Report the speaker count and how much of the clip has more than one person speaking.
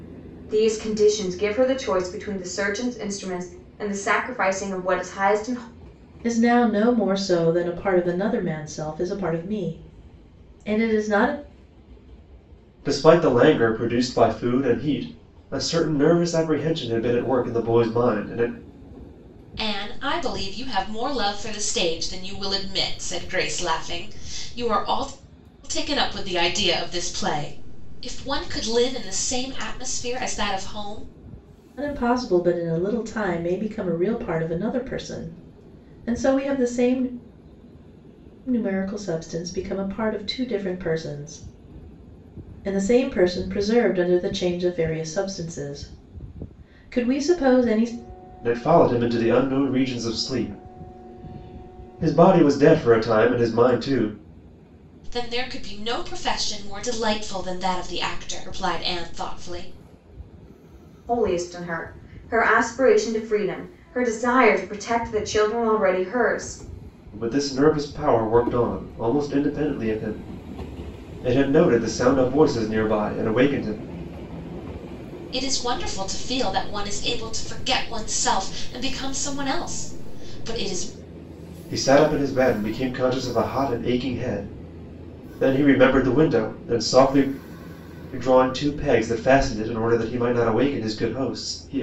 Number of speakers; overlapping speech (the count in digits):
4, no overlap